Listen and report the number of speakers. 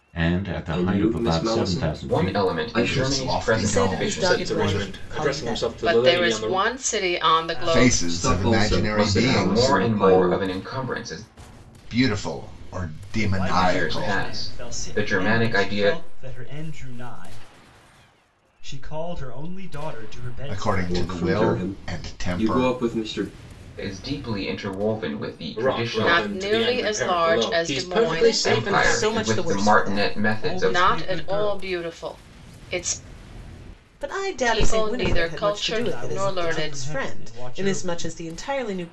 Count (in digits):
8